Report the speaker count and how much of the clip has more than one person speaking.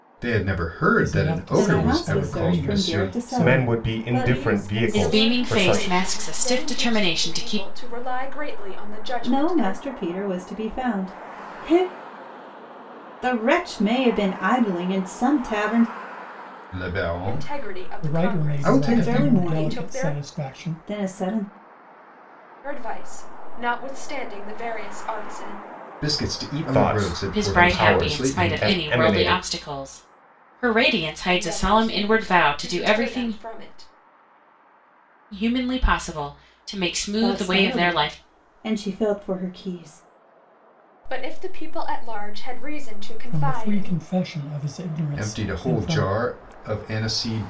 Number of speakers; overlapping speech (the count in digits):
6, about 39%